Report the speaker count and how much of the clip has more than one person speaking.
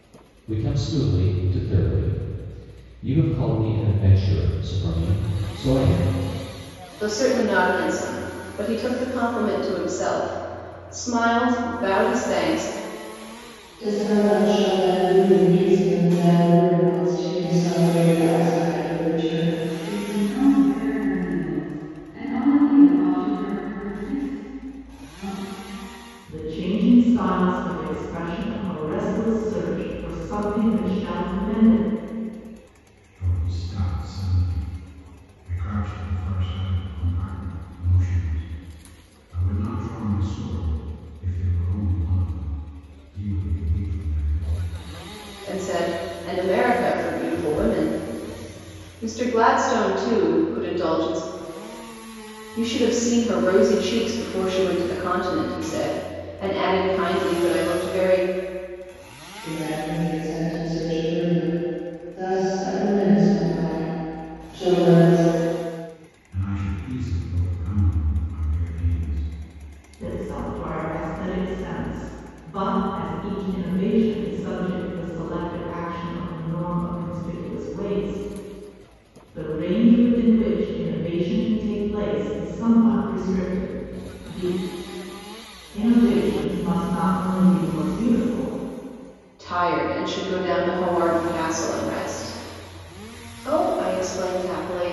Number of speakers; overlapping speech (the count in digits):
6, no overlap